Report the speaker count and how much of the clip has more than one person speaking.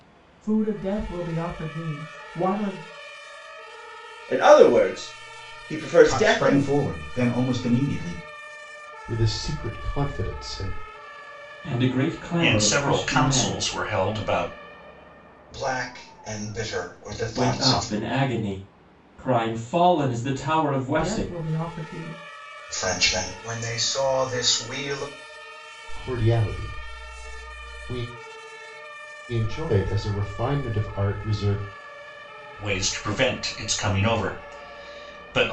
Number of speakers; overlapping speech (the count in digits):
7, about 8%